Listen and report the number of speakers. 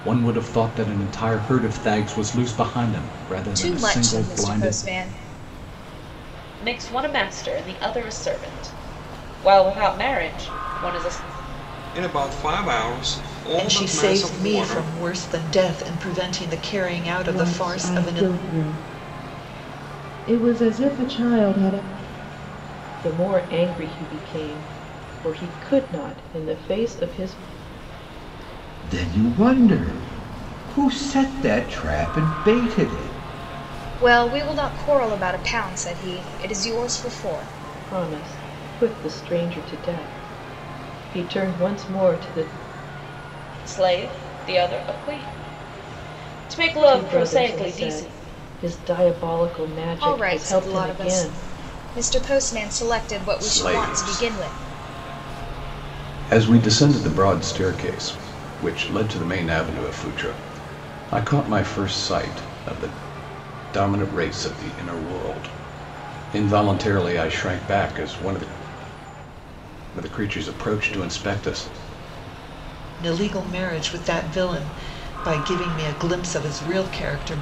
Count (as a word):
eight